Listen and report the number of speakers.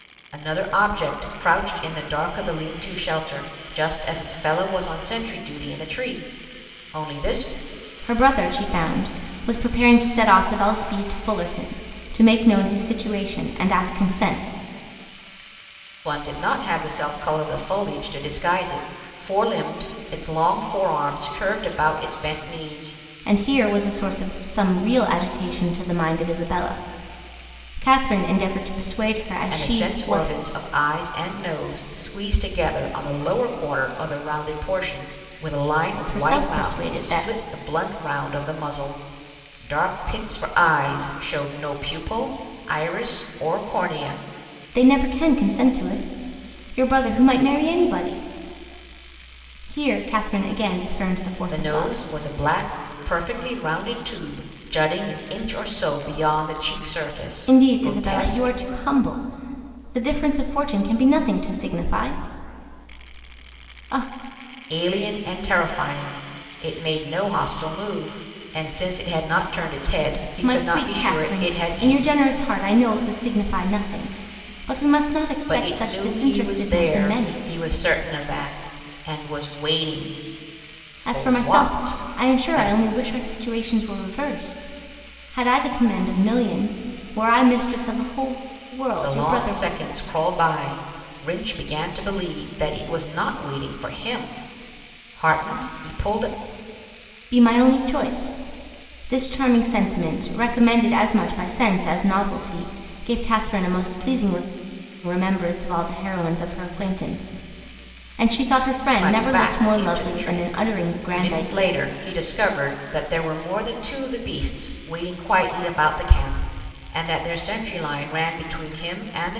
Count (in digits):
2